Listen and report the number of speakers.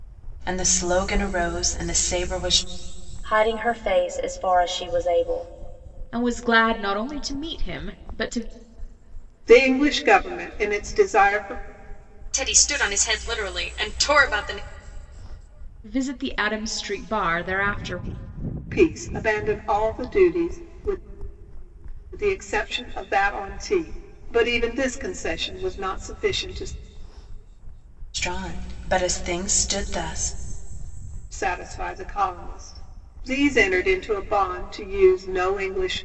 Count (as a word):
five